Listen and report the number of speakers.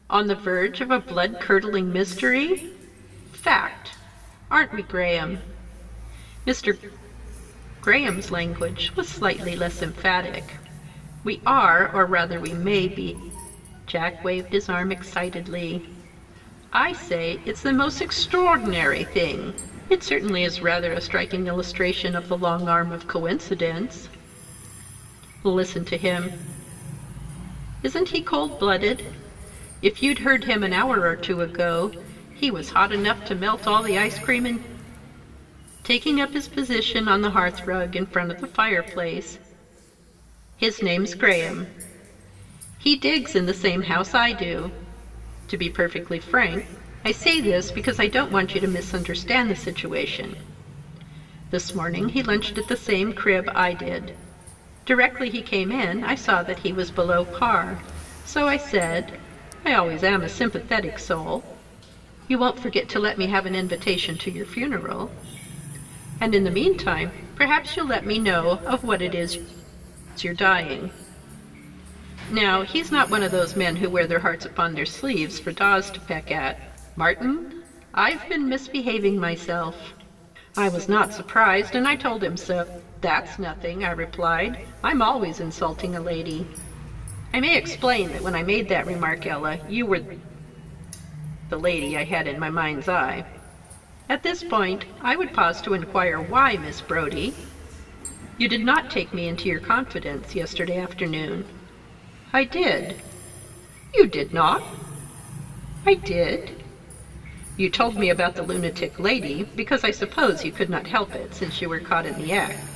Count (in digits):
1